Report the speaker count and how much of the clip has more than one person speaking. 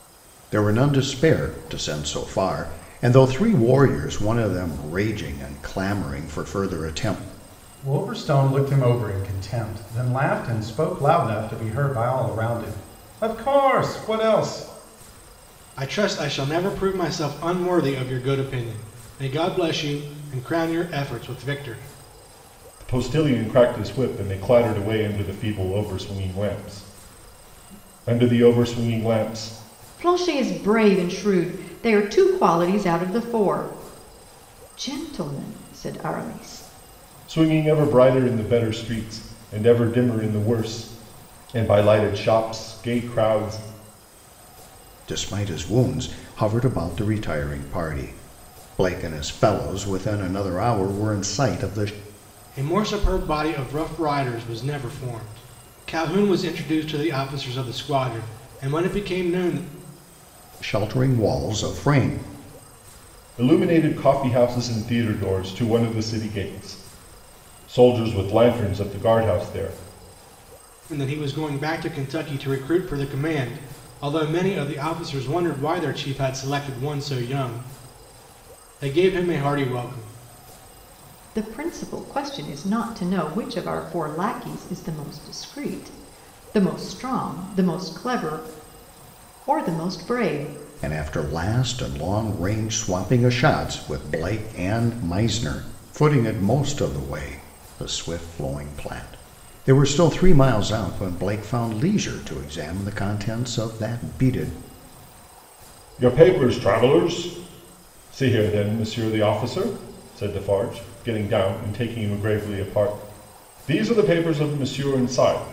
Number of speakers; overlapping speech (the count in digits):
5, no overlap